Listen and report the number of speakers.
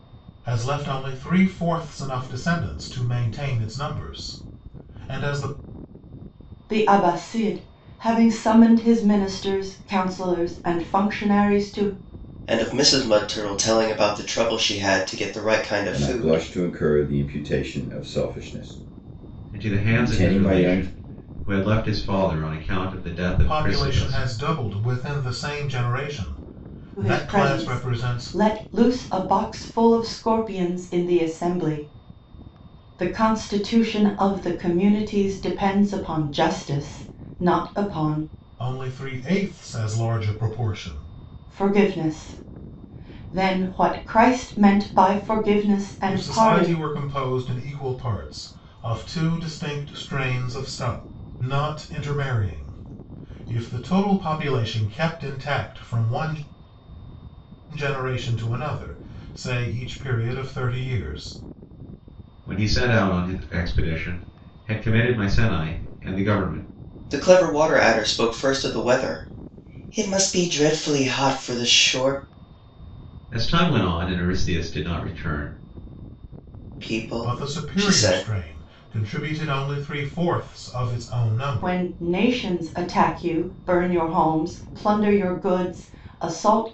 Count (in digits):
5